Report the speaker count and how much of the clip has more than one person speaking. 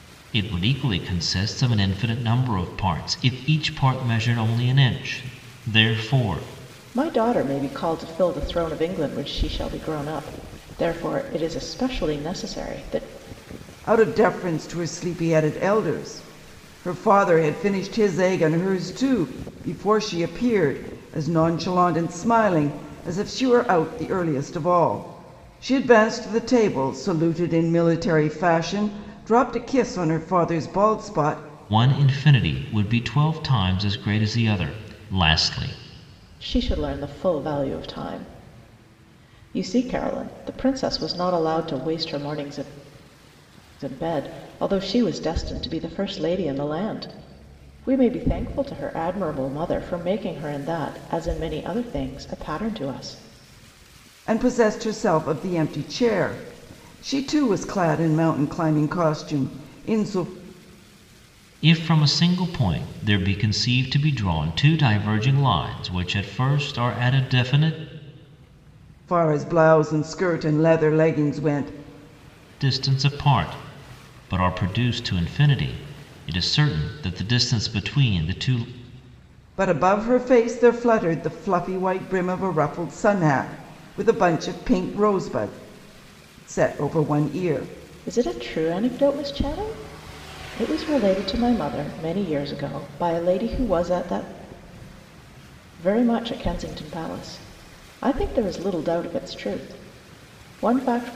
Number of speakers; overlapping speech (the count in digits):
3, no overlap